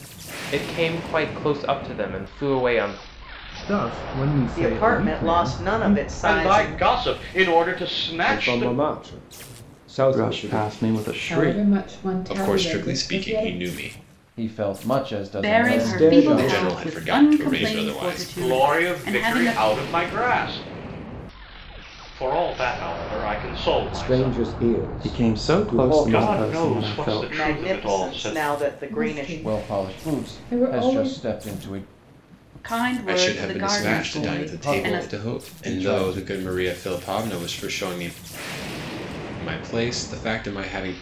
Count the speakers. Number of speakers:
10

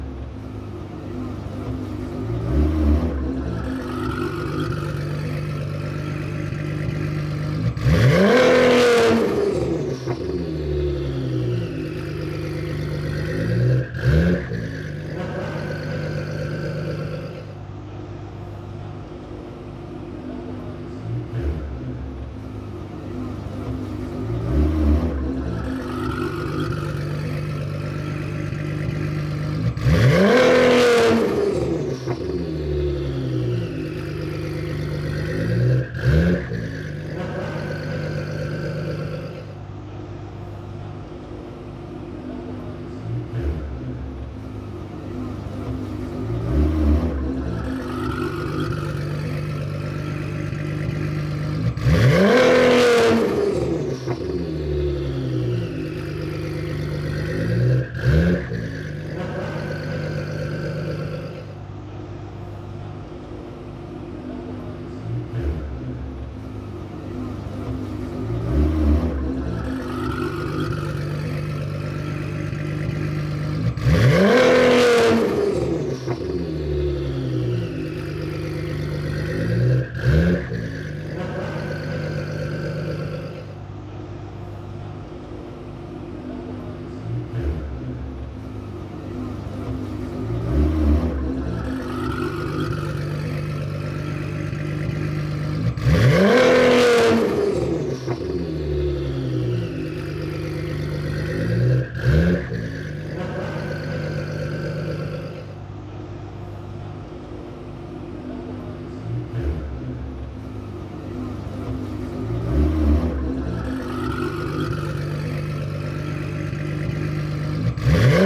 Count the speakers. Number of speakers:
0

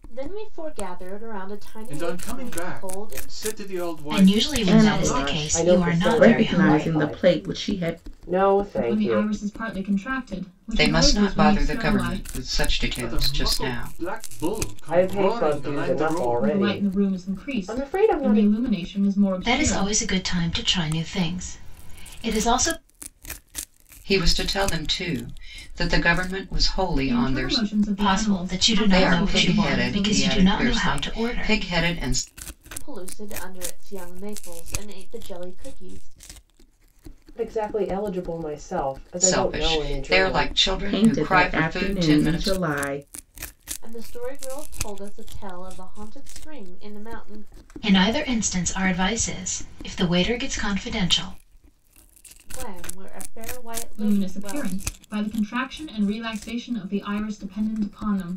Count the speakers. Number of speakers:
7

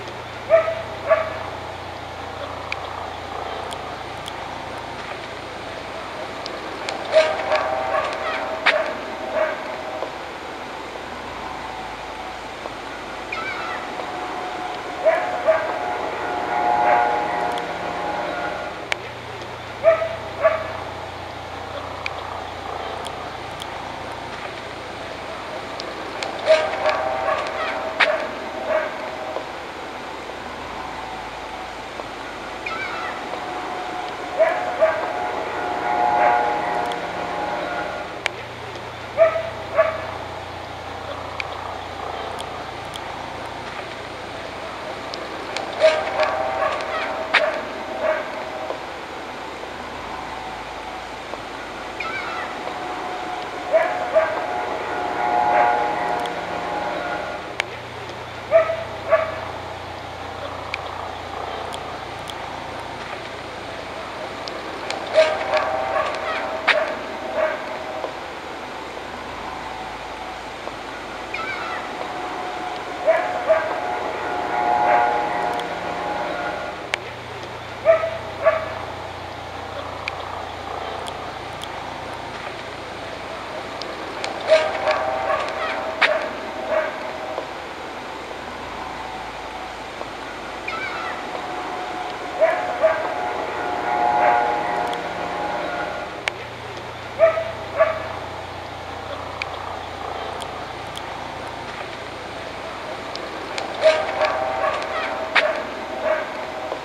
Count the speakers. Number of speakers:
0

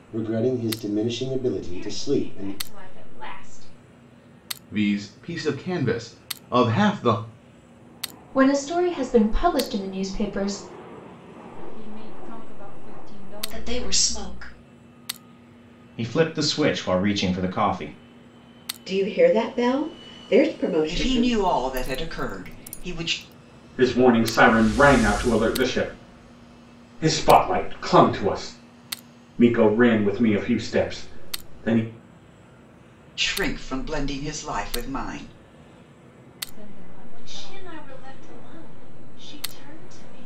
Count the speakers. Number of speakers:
10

